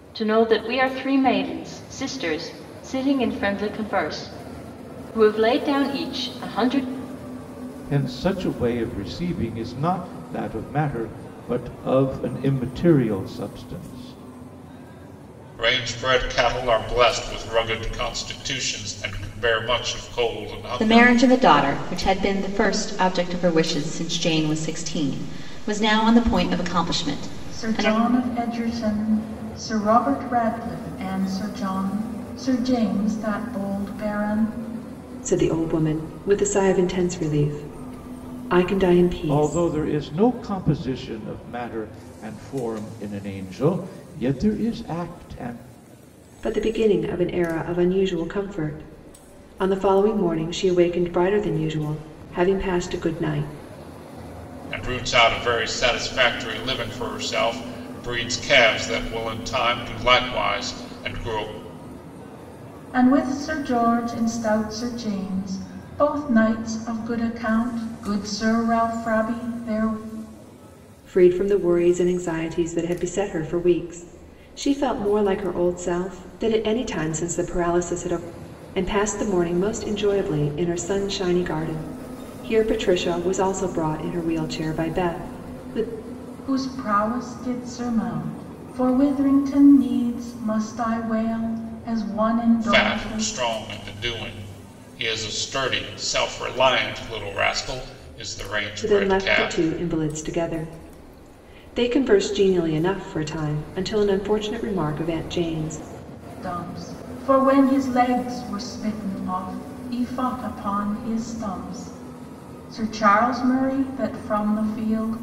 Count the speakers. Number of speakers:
six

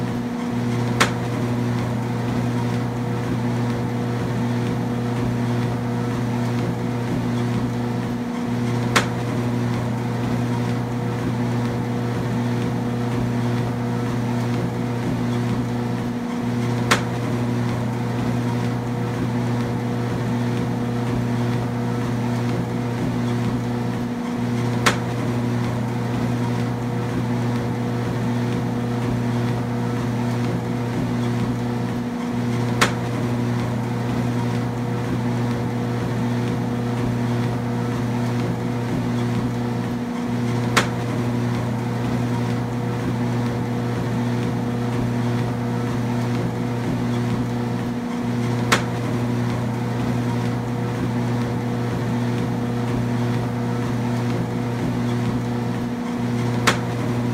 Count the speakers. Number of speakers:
zero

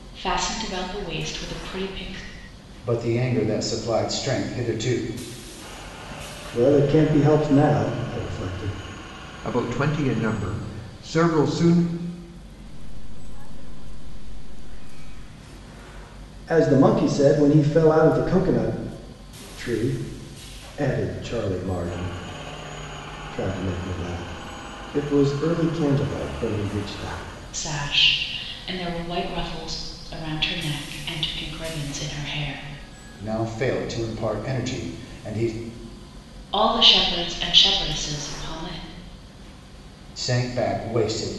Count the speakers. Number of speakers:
five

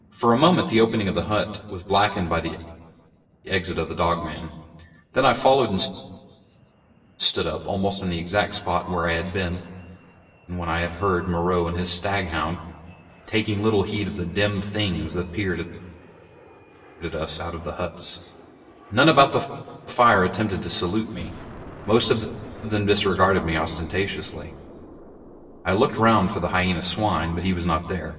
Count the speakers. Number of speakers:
one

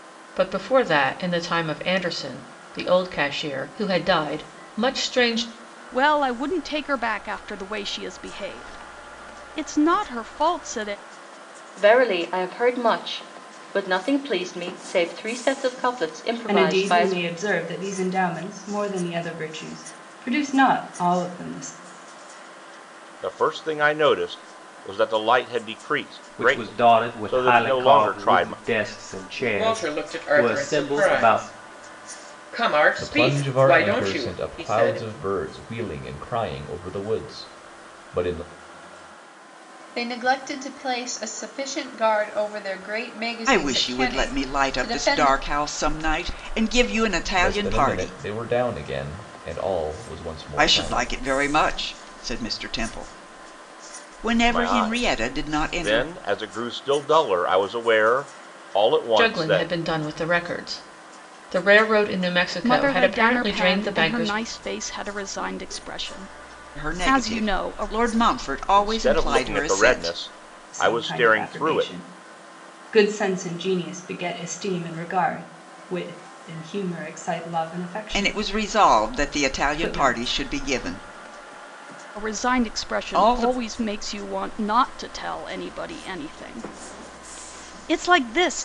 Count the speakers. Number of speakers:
ten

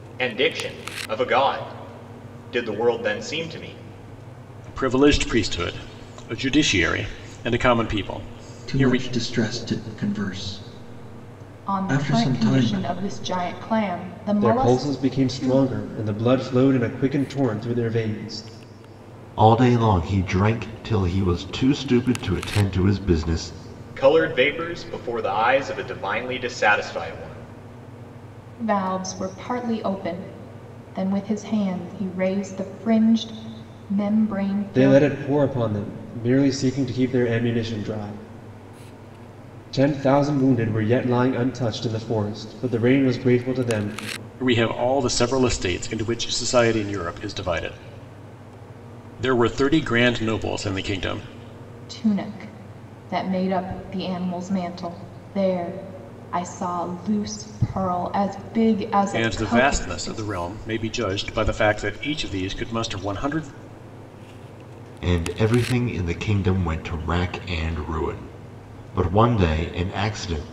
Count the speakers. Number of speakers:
six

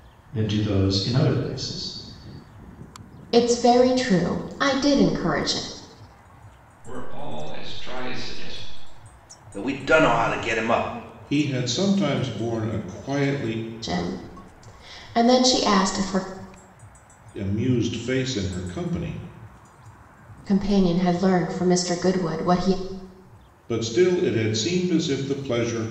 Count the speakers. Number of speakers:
five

